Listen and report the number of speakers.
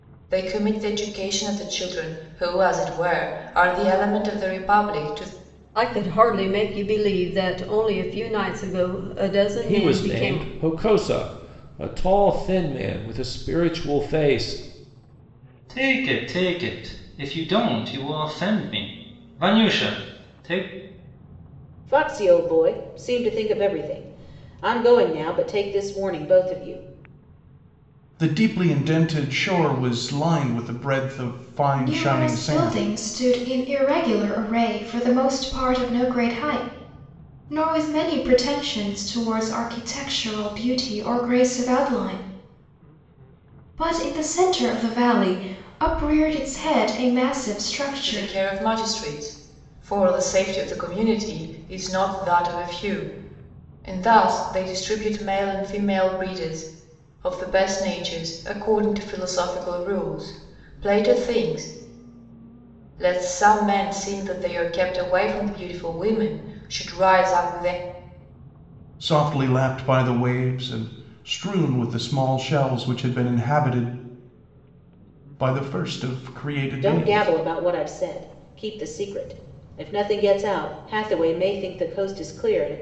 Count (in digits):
7